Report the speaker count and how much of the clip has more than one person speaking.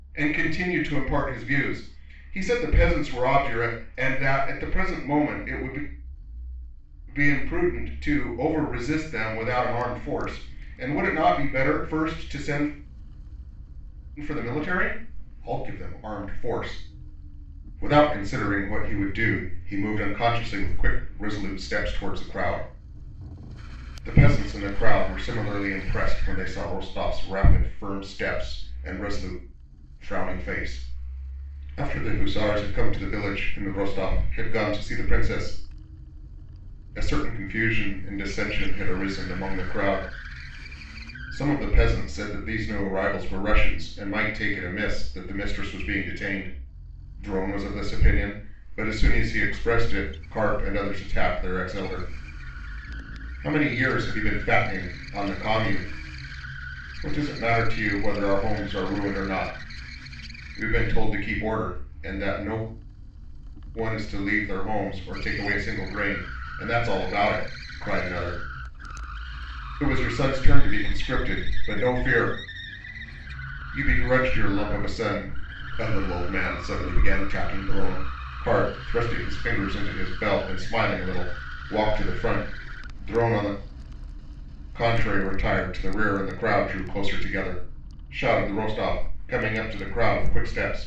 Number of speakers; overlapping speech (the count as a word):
one, no overlap